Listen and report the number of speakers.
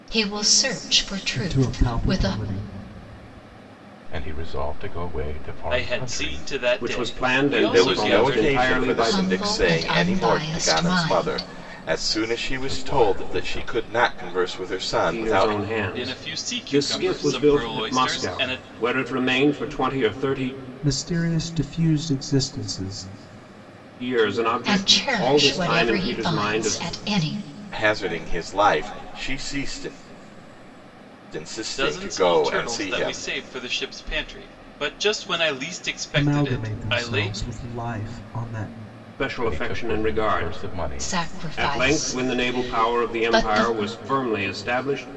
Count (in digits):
6